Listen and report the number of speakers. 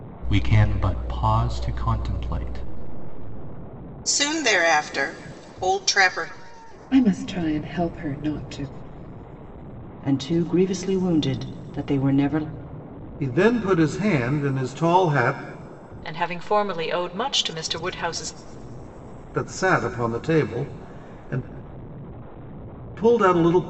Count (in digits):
6